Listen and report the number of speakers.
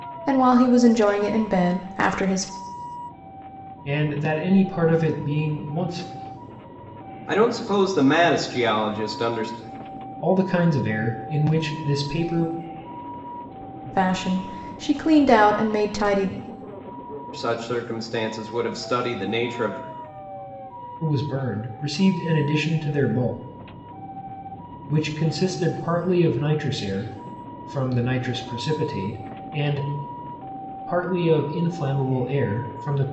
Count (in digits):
3